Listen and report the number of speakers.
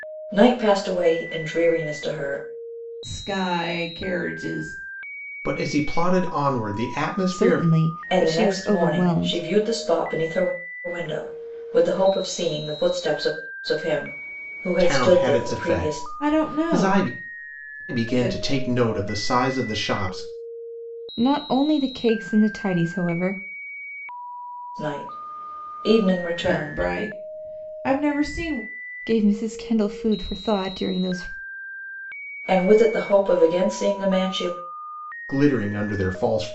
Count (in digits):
4